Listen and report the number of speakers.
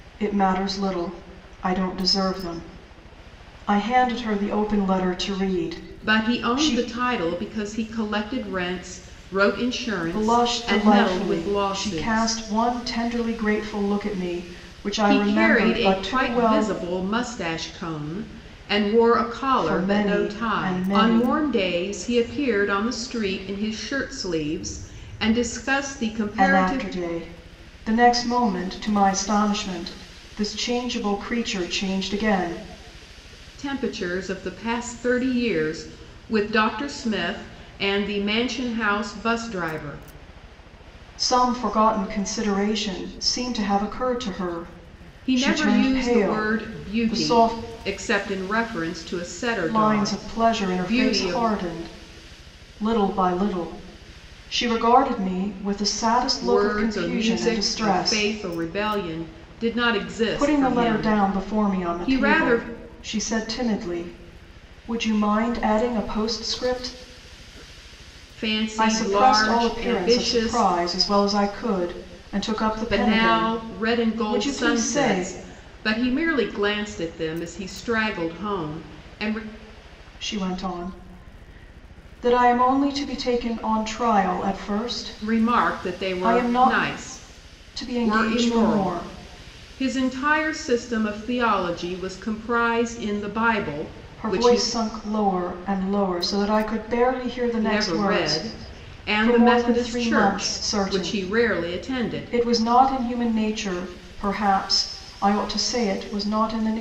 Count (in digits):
2